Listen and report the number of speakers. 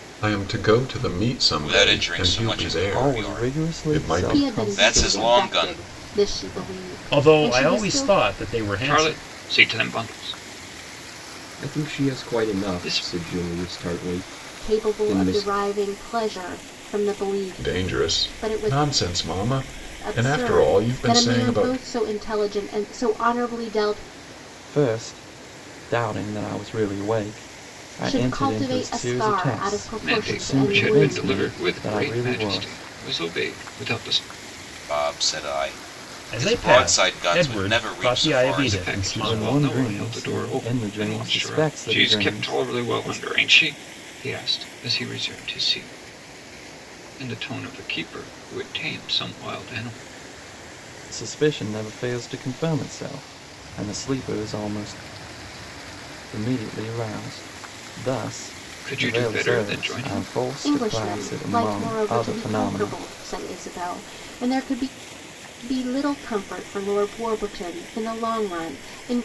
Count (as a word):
seven